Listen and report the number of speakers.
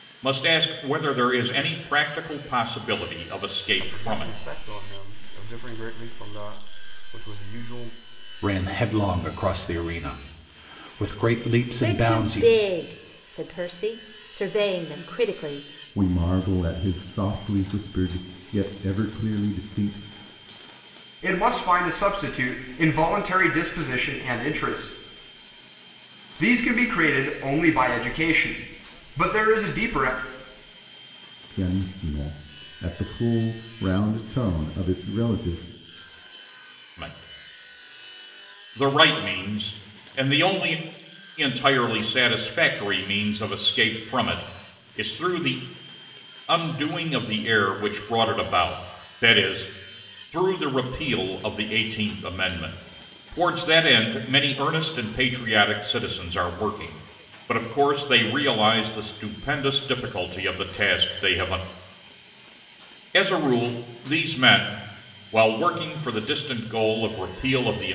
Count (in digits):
6